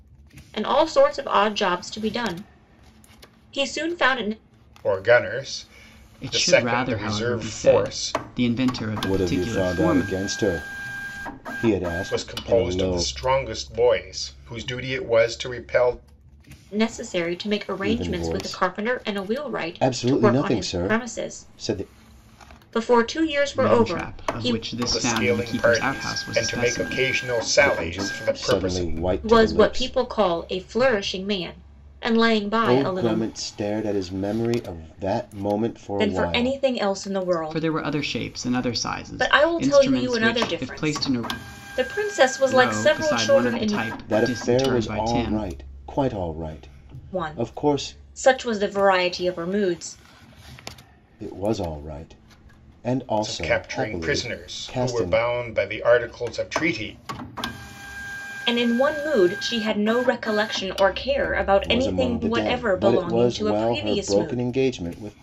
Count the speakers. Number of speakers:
4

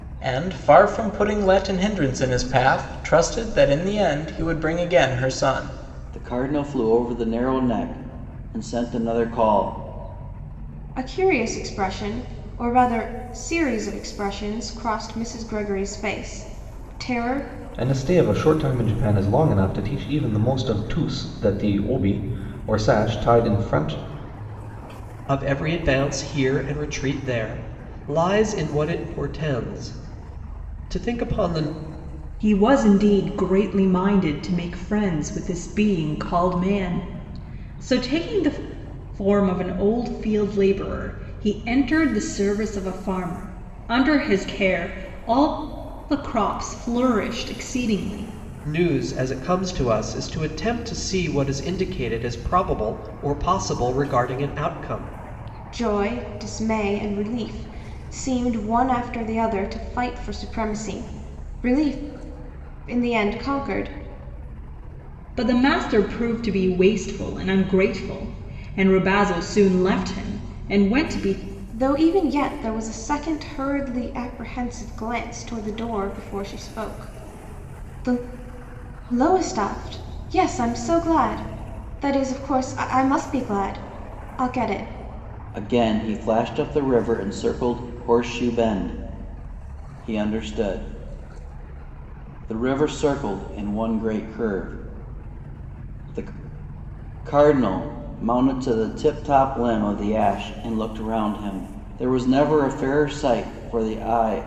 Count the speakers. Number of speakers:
6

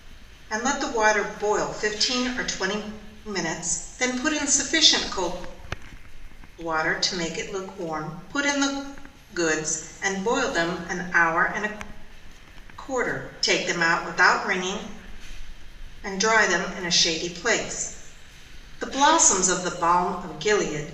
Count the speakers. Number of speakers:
1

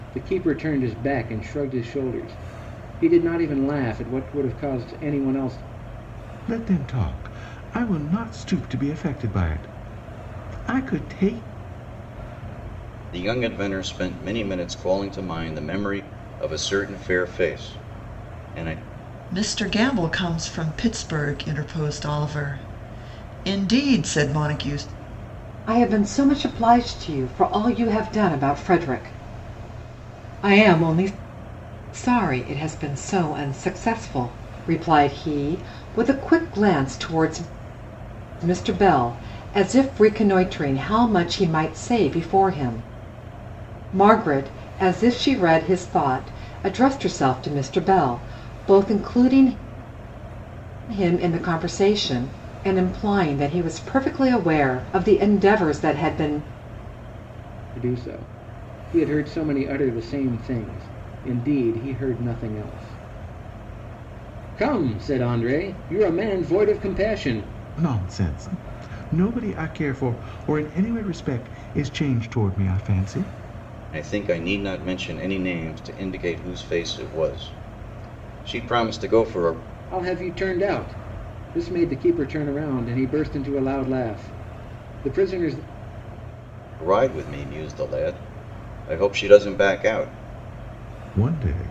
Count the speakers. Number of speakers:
5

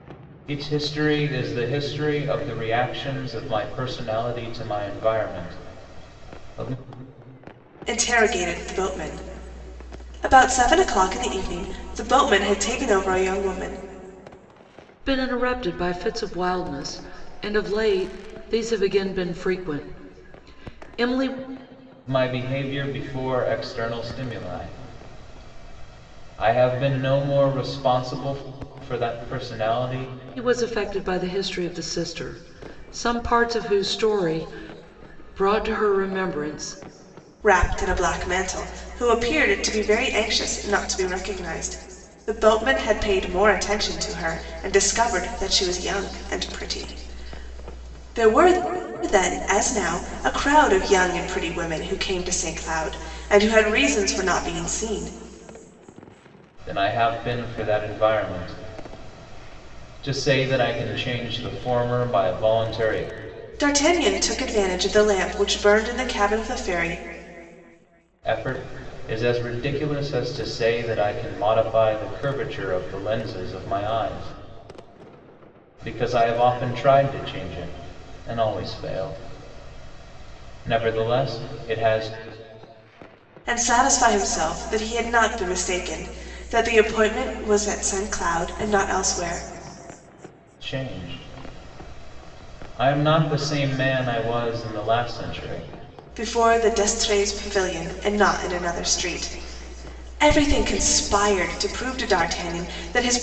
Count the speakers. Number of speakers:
3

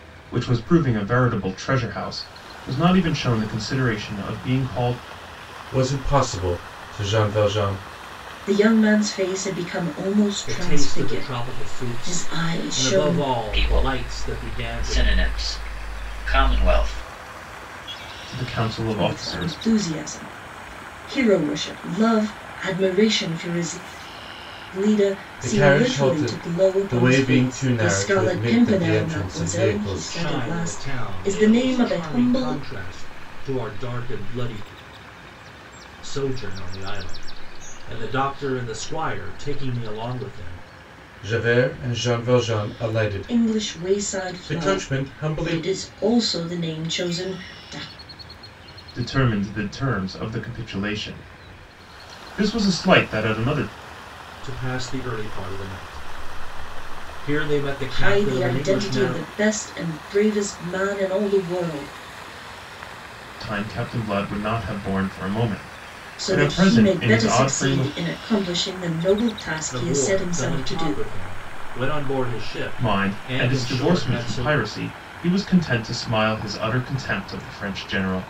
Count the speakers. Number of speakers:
5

